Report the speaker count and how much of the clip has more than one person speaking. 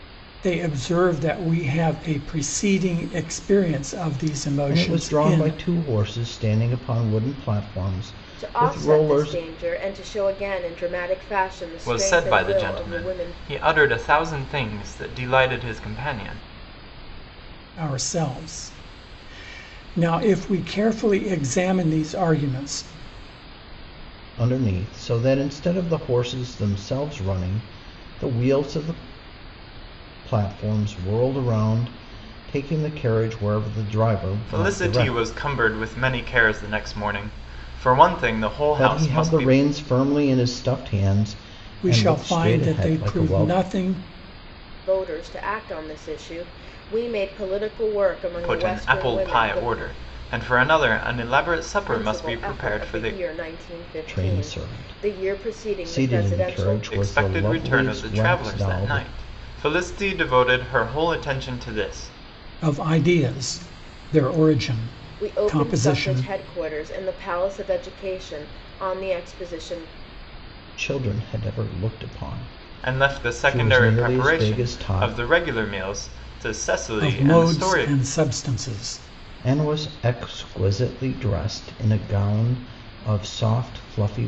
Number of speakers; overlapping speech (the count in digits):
4, about 23%